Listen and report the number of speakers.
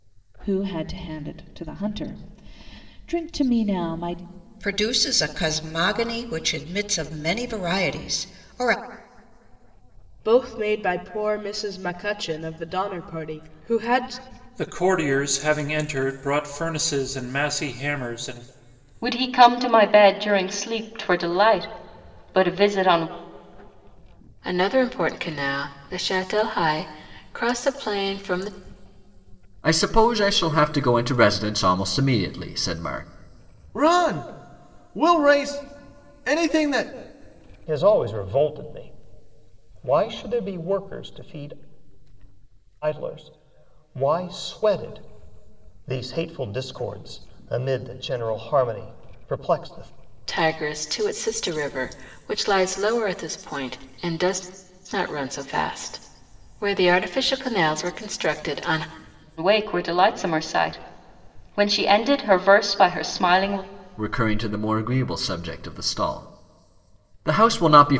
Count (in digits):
9